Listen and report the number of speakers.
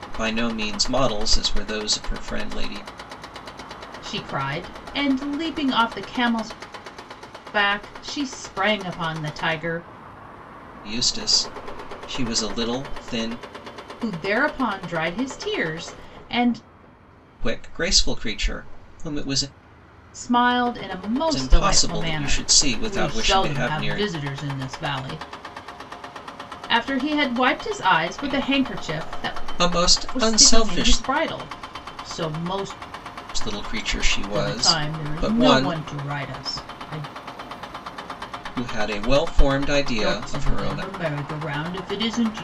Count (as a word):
two